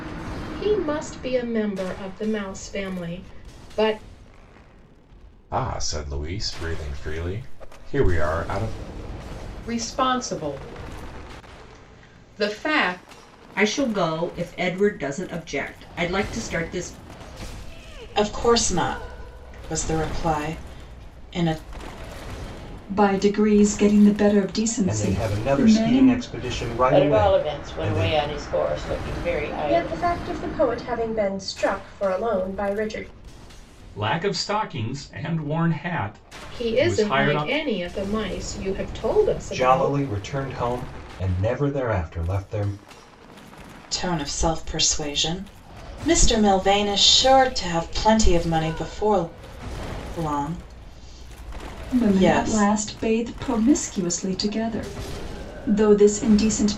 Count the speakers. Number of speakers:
ten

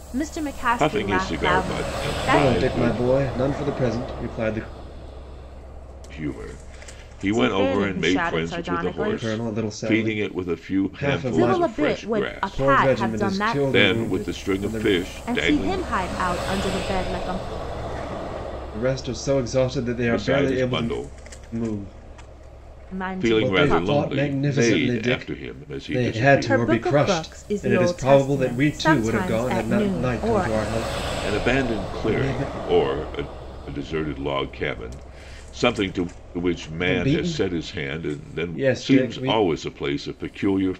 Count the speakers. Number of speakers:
three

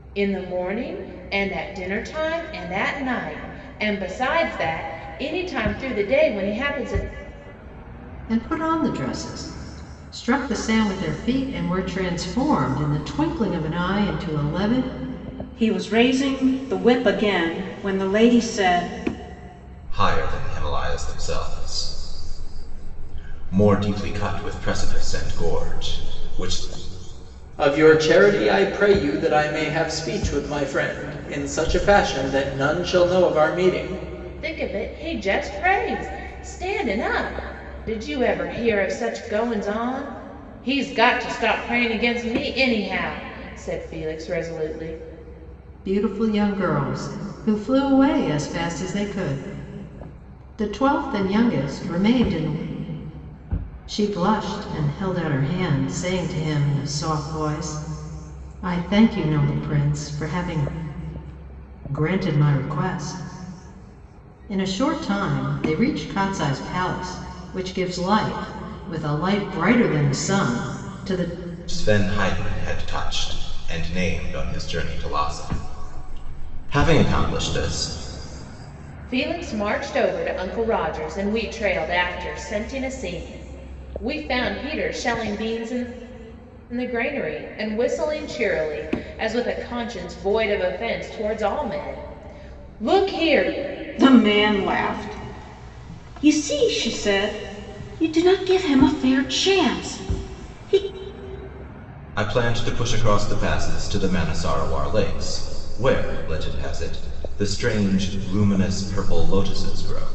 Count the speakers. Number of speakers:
five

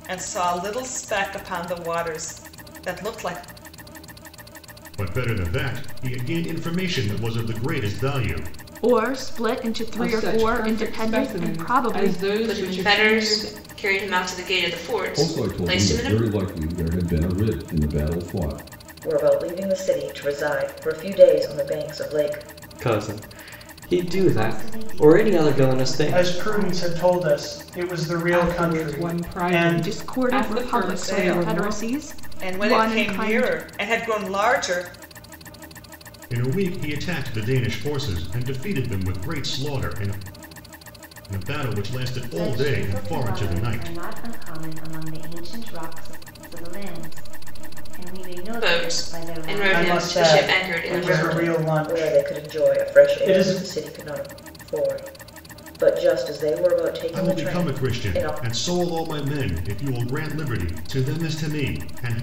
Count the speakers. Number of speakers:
ten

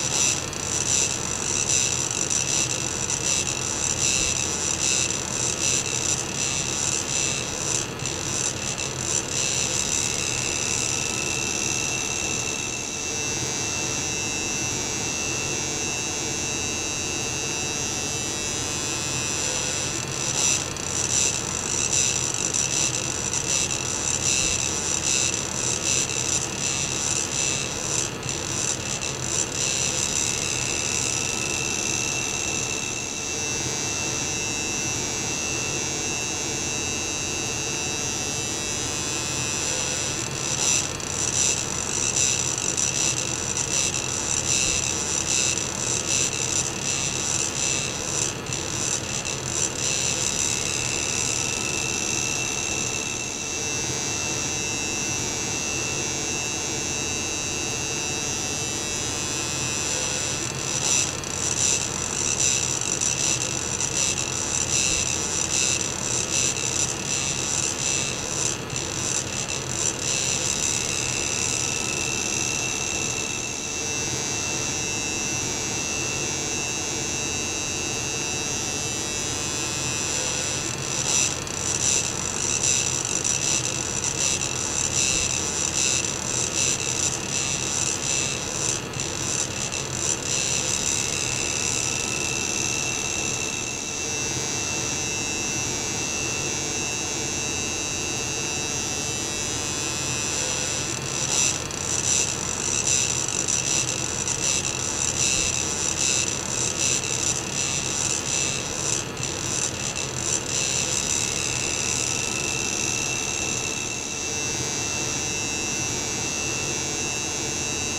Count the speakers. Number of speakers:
zero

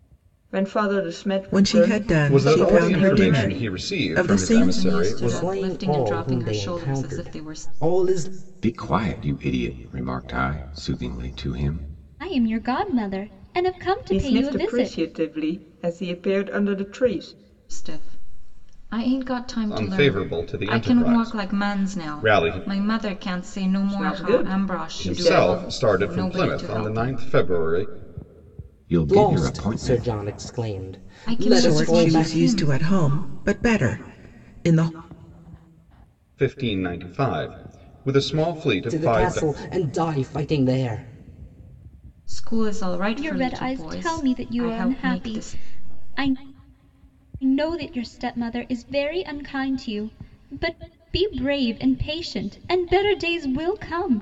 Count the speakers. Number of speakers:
seven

